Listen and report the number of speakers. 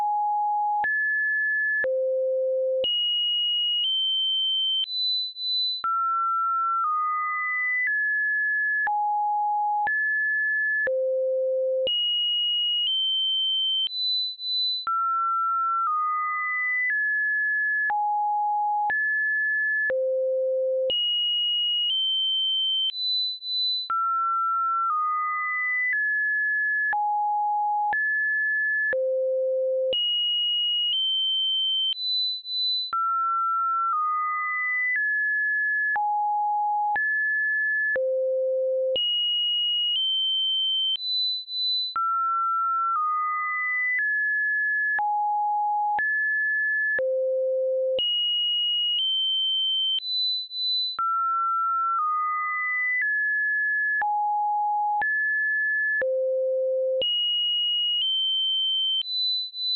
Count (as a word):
zero